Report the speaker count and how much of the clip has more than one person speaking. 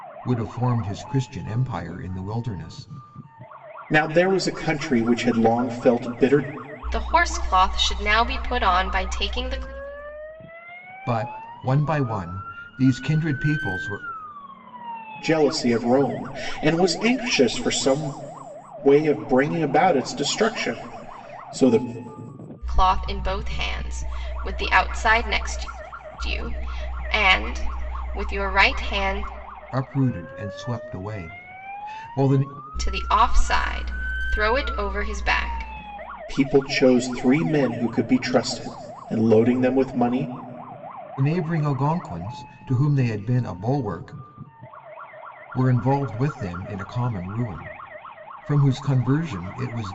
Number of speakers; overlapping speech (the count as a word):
three, no overlap